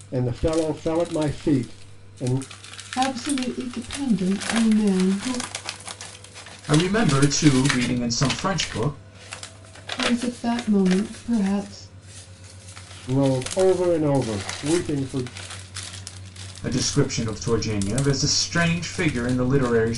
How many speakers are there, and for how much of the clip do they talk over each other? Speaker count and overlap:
3, no overlap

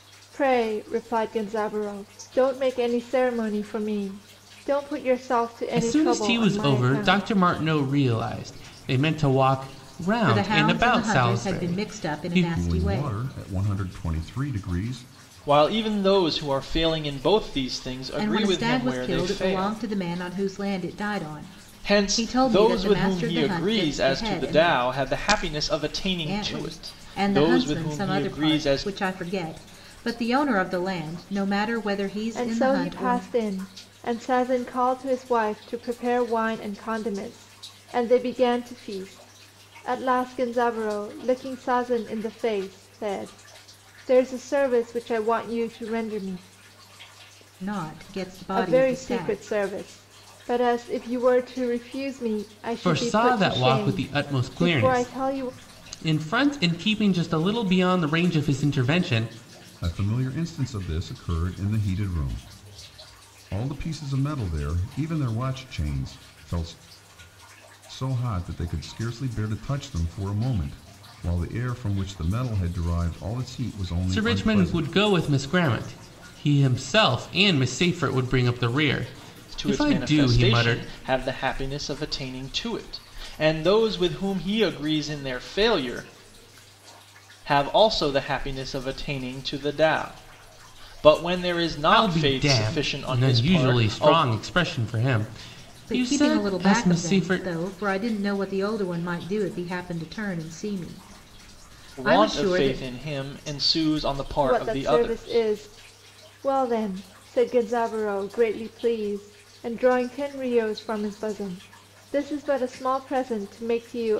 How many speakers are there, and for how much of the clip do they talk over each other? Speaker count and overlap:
5, about 22%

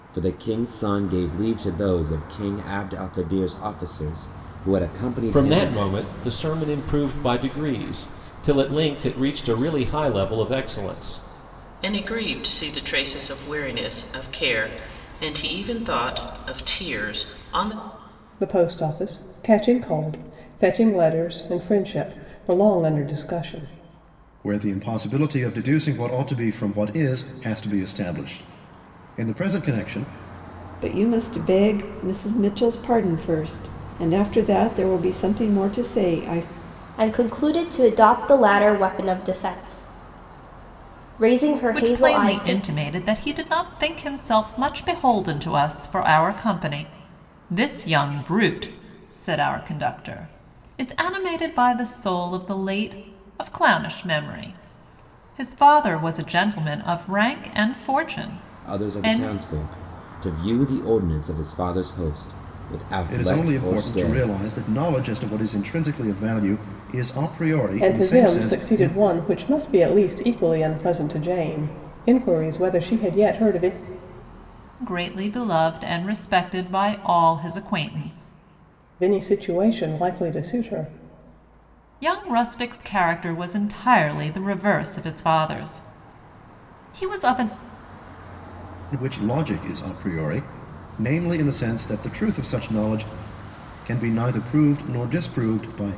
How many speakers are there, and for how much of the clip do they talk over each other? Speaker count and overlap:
8, about 5%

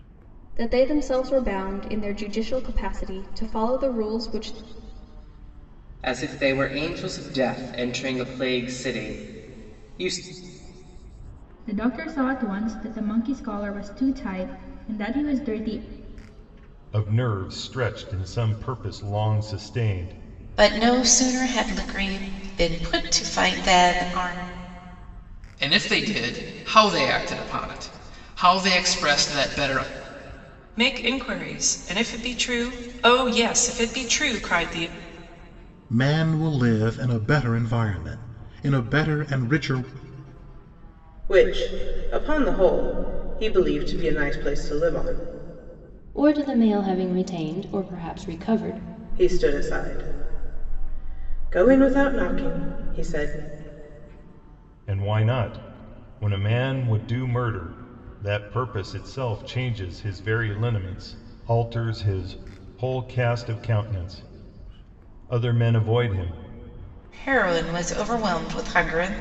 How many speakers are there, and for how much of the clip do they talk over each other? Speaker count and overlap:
10, no overlap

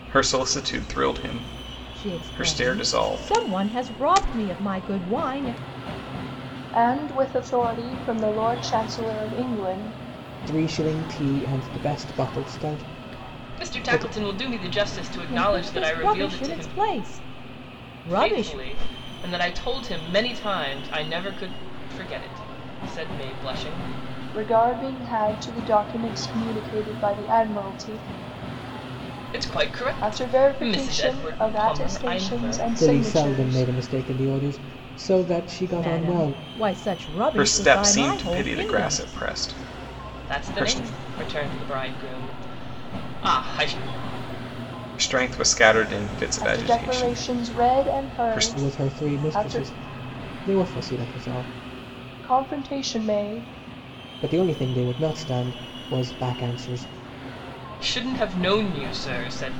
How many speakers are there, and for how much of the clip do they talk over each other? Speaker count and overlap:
5, about 23%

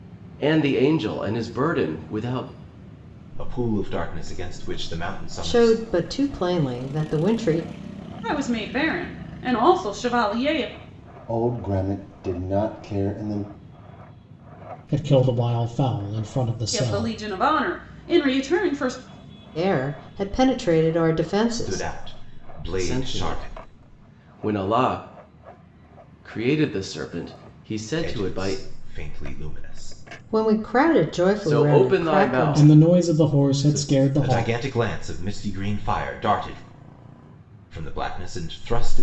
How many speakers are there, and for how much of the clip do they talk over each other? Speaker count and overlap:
6, about 14%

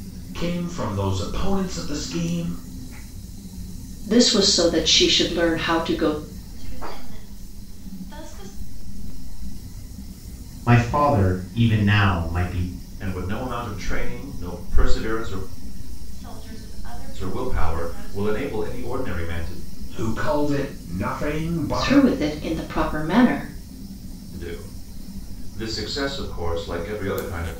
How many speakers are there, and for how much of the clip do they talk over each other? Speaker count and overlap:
6, about 23%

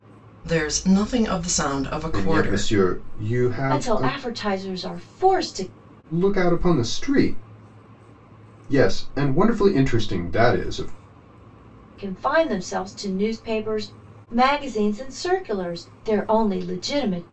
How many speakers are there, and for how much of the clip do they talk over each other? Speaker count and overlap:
3, about 6%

